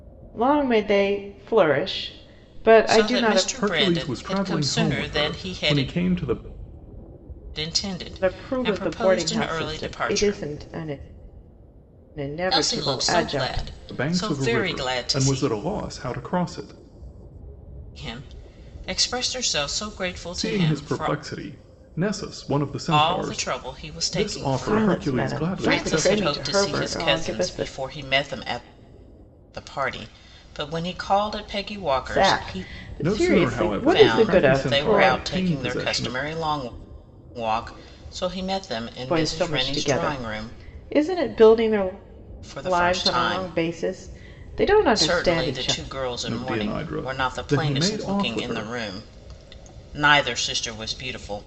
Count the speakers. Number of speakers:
three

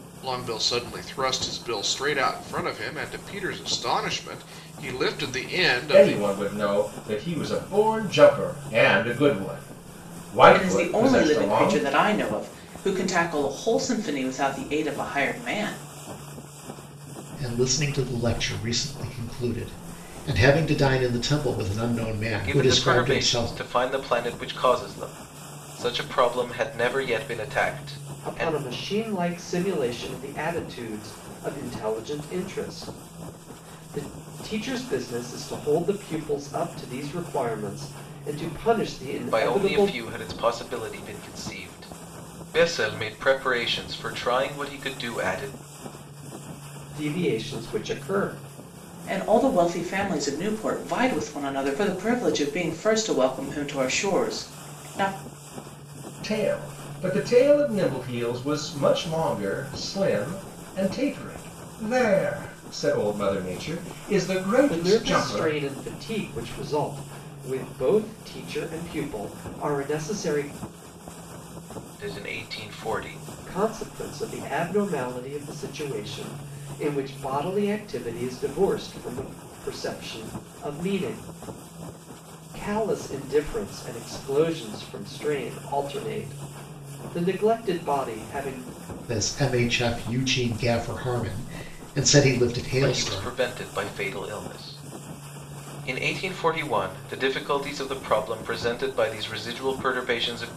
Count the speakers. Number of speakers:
six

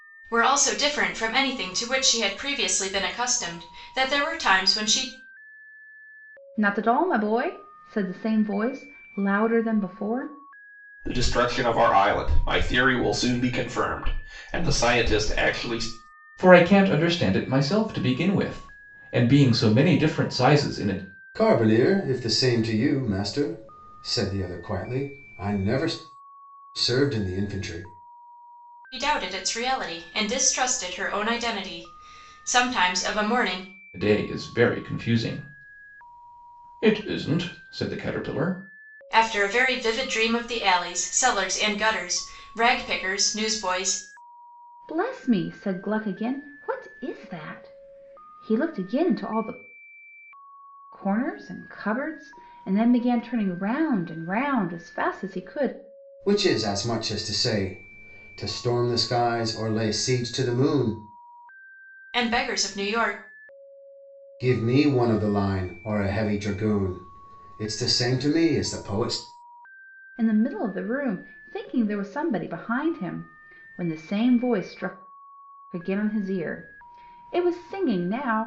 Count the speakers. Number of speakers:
five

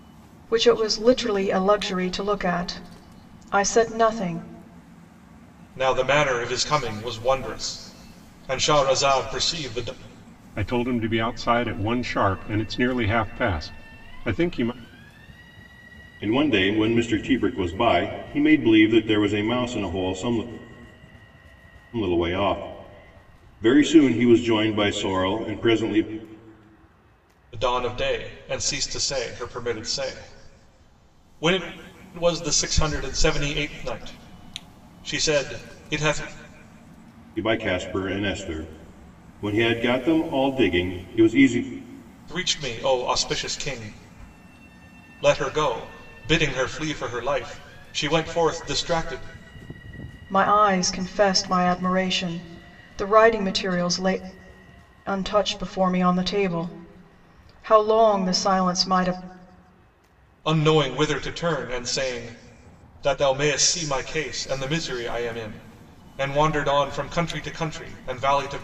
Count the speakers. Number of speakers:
four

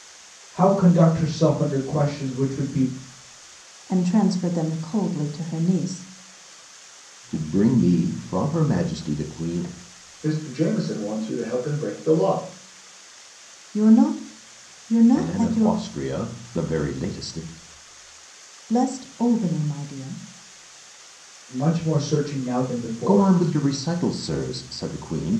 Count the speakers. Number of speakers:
four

